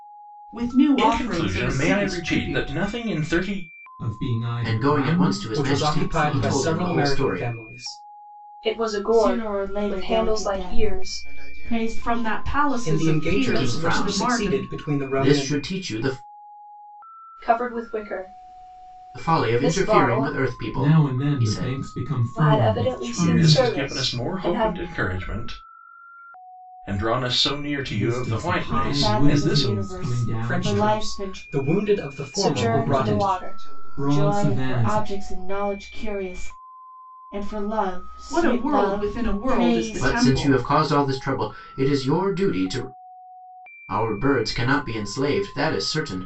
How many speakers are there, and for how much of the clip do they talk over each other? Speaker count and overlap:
eight, about 54%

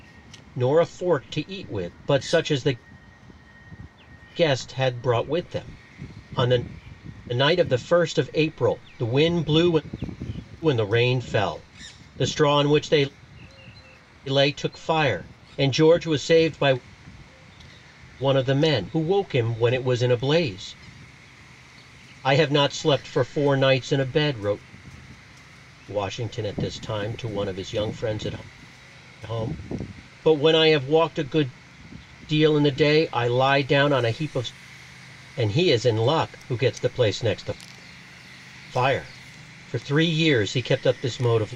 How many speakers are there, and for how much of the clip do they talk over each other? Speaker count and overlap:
one, no overlap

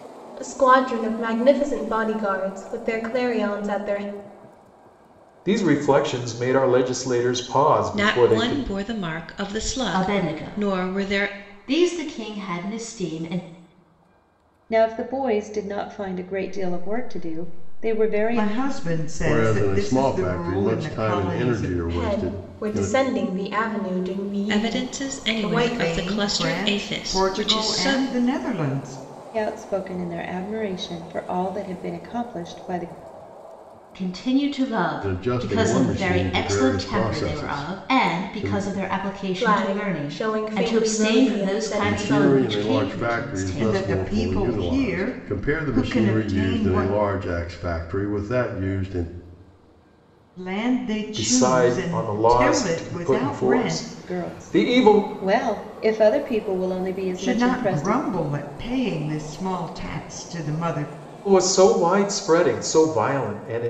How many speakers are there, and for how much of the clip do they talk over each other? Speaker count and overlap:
eight, about 44%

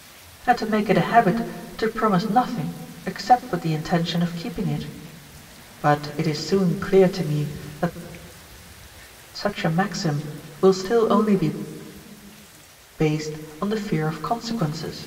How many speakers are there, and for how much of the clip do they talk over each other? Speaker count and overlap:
one, no overlap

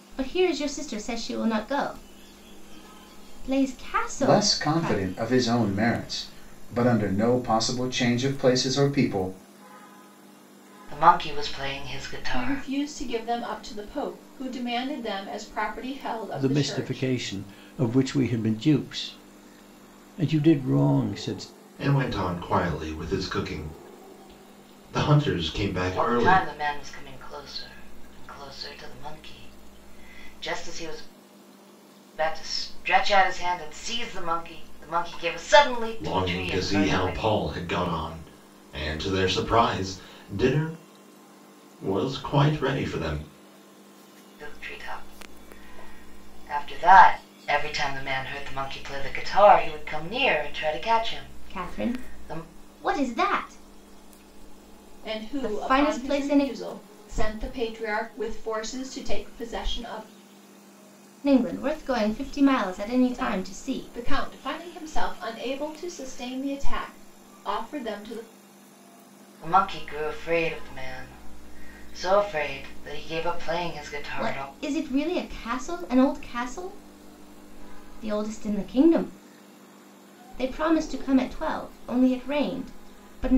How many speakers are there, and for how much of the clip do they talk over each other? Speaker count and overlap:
six, about 9%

